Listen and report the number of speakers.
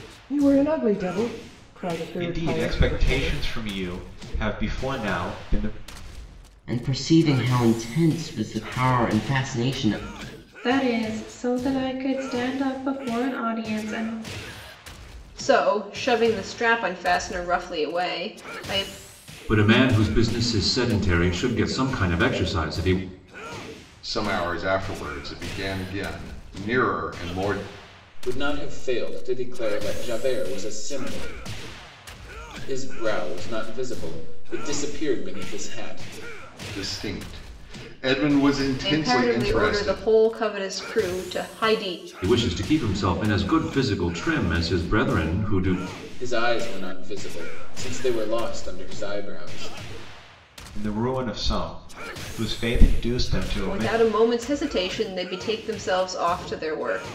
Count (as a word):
eight